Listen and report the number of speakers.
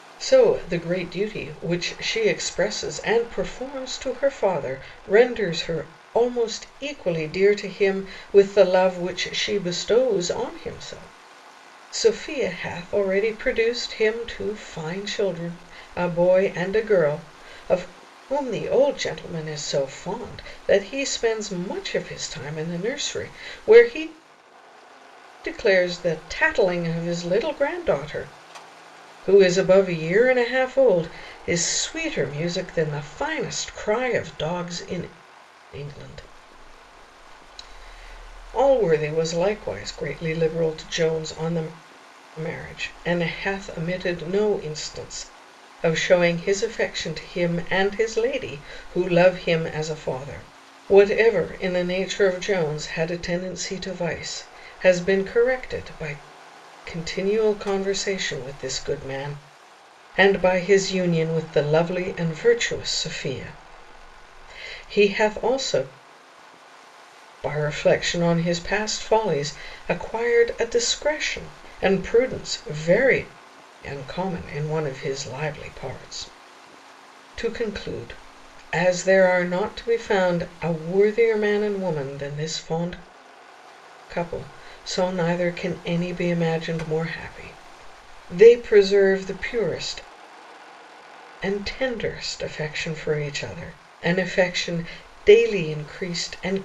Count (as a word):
one